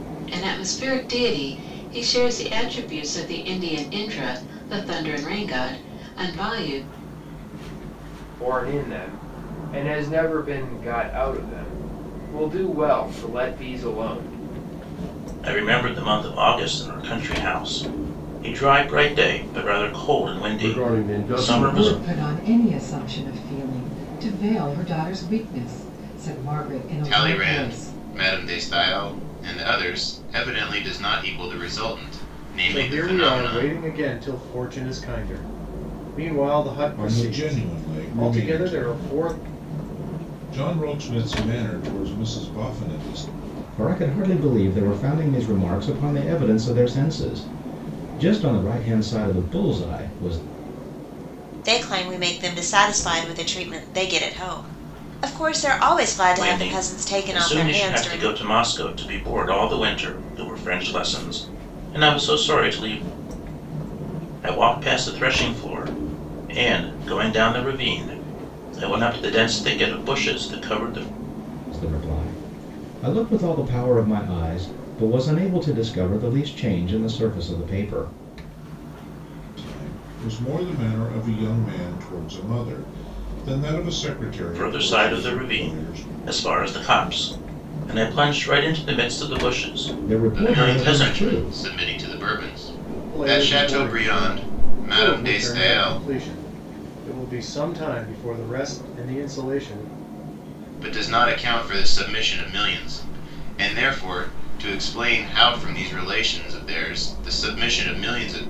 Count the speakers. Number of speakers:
ten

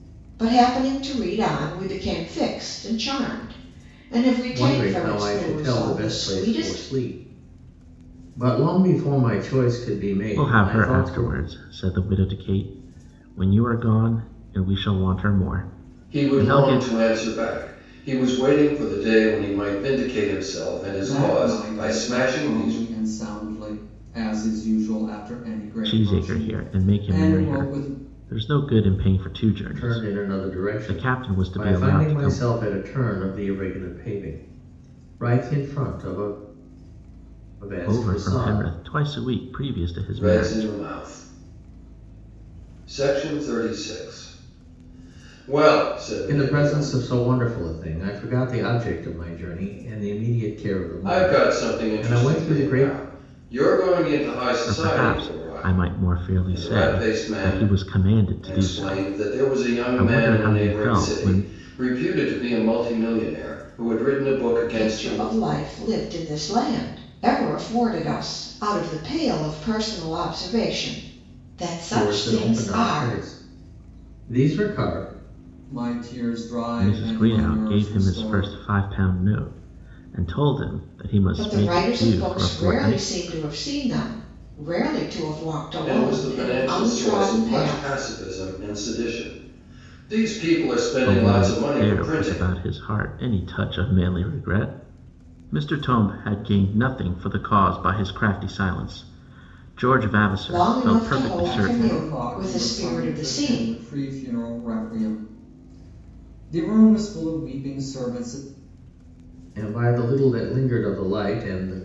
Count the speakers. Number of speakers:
five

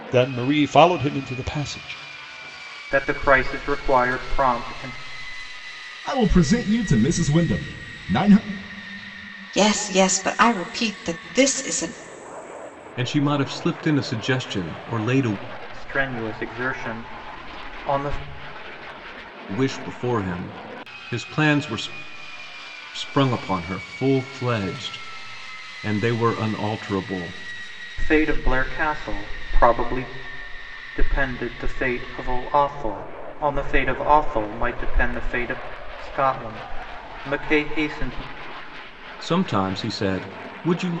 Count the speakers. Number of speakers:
five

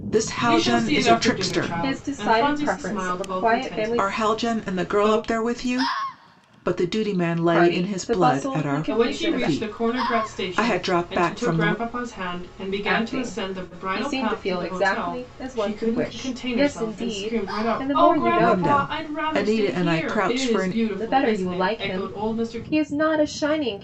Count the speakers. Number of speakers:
three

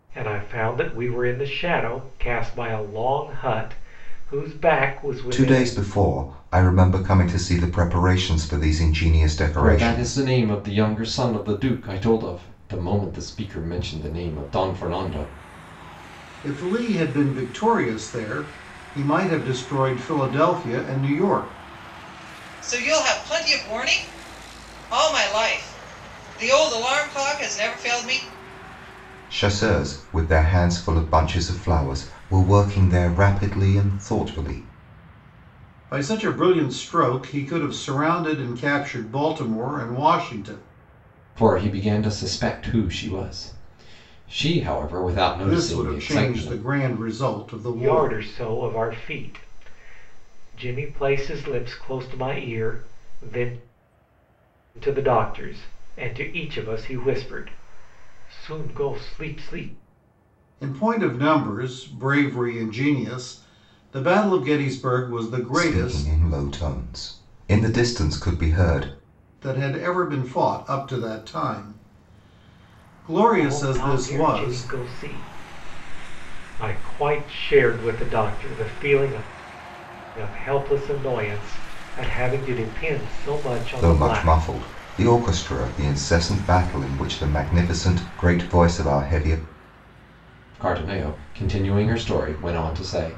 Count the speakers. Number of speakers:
five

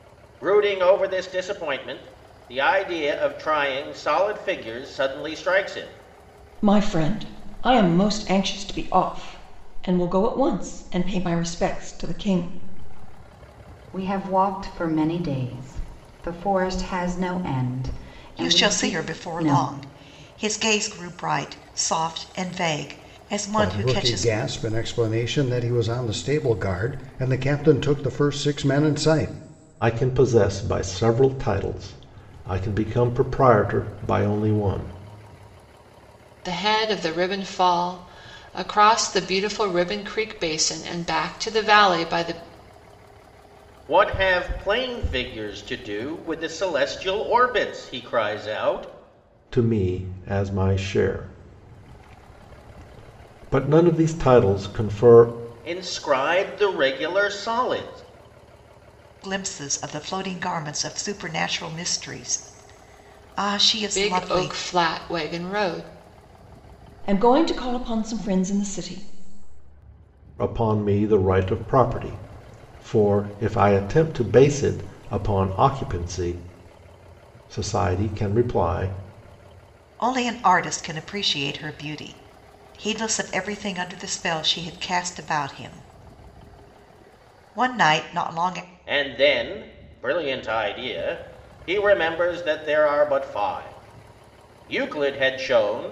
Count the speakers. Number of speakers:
seven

